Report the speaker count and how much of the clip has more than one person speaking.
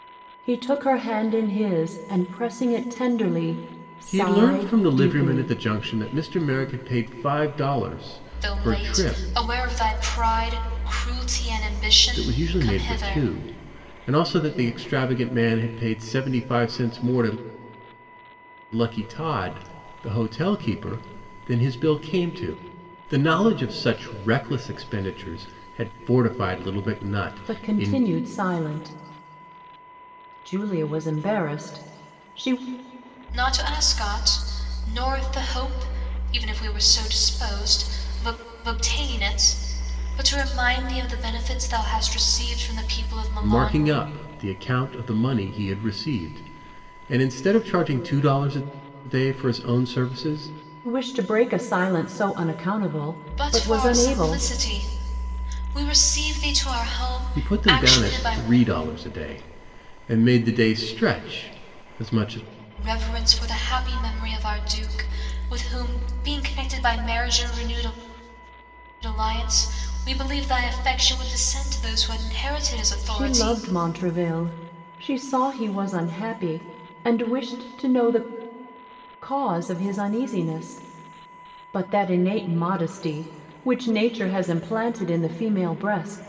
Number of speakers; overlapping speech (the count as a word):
three, about 9%